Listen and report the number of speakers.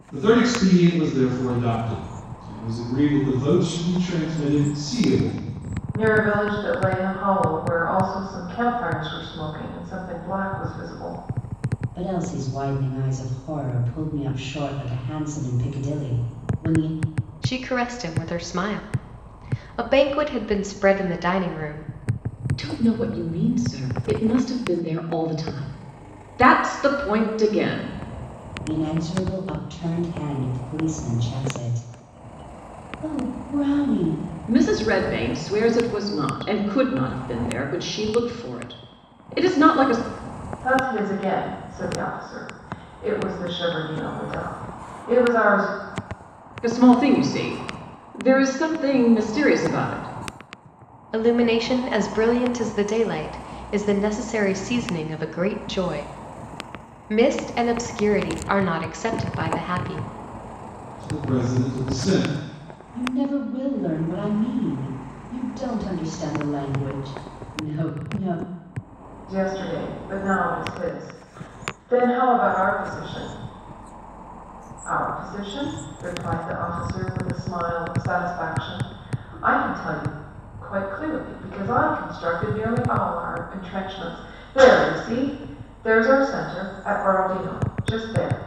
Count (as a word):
five